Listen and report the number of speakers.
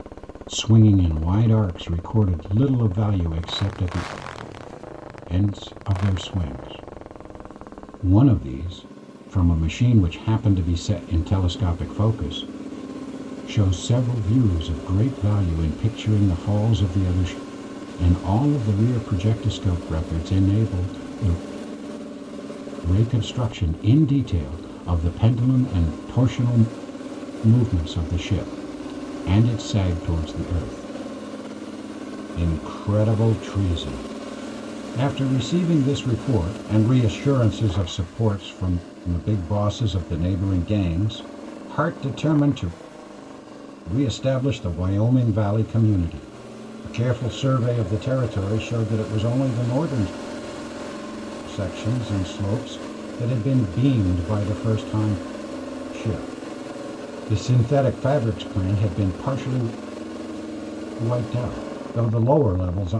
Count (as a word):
one